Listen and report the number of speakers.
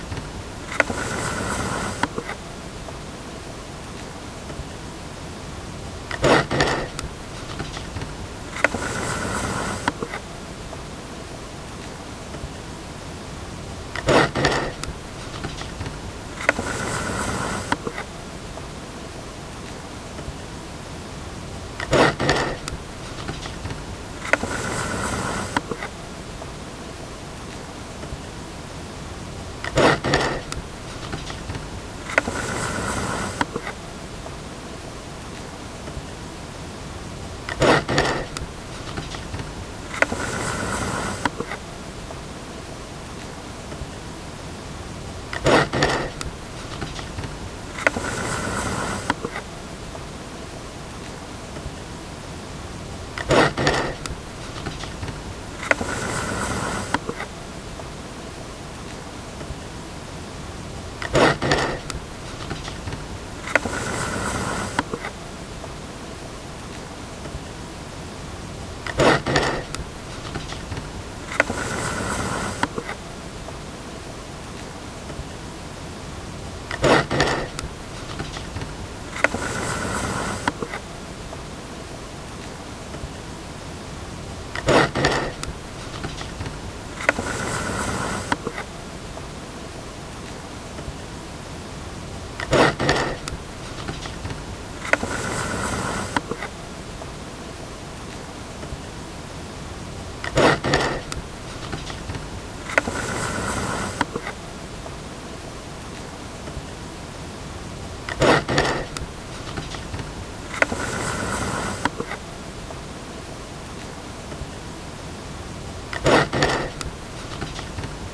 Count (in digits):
0